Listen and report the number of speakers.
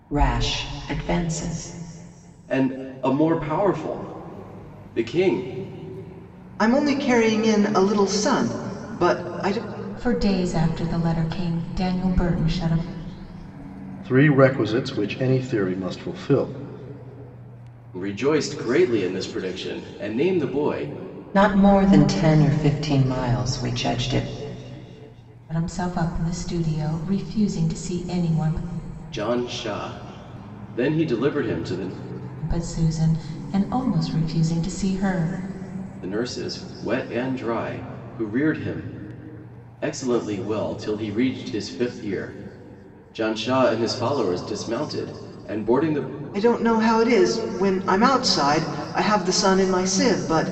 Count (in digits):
5